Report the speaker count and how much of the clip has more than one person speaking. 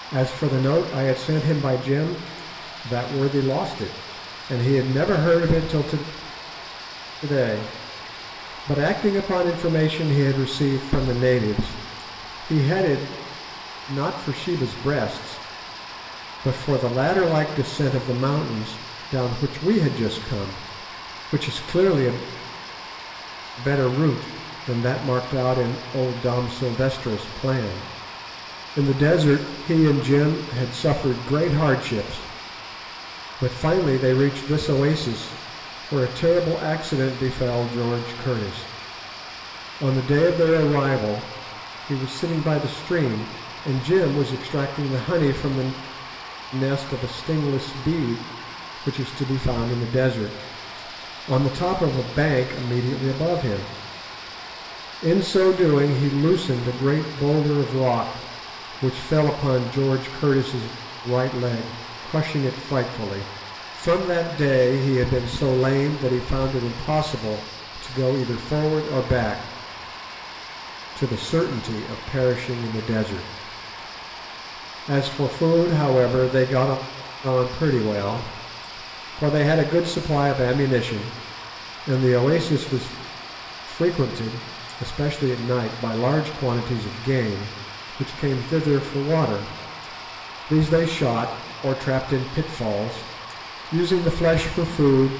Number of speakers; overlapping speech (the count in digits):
1, no overlap